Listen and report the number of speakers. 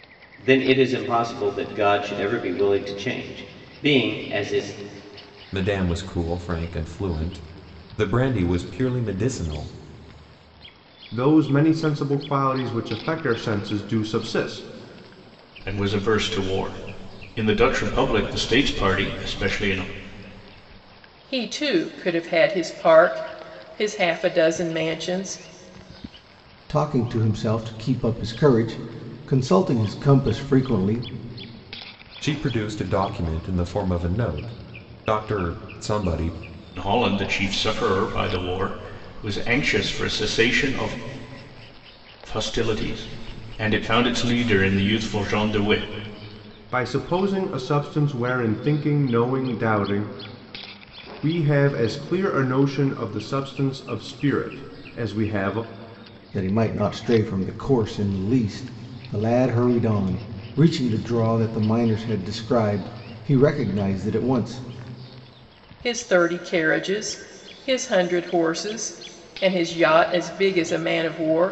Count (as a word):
six